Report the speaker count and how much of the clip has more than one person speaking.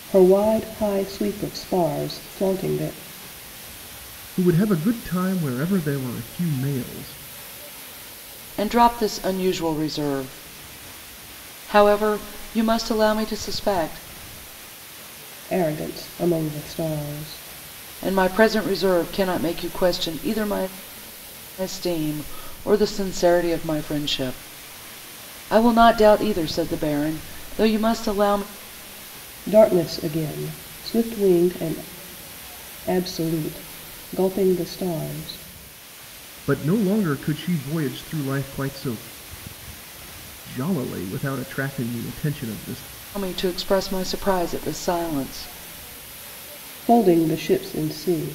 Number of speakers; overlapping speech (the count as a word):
three, no overlap